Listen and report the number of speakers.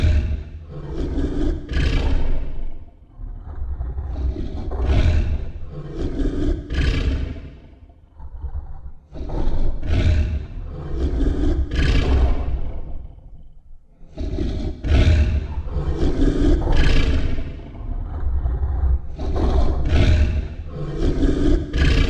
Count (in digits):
0